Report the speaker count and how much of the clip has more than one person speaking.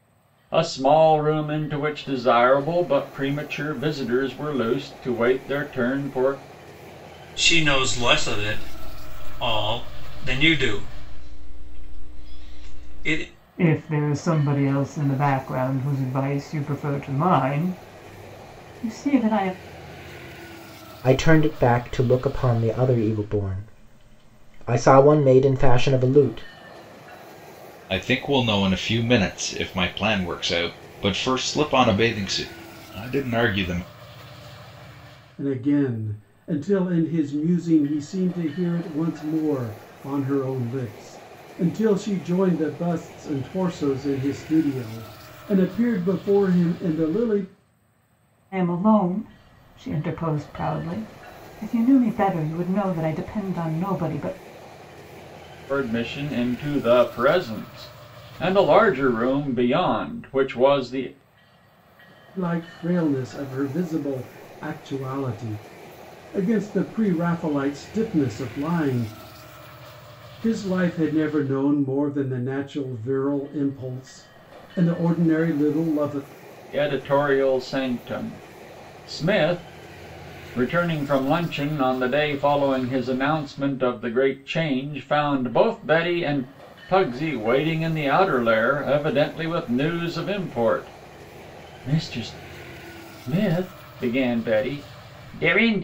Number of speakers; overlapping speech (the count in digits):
6, no overlap